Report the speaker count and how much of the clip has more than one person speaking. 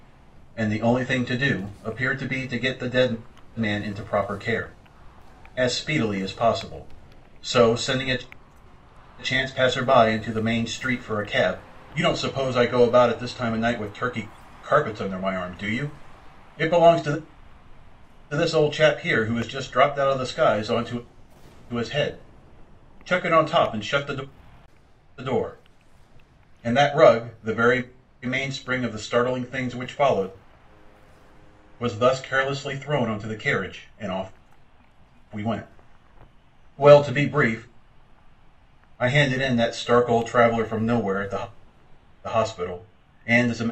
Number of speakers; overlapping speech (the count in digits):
1, no overlap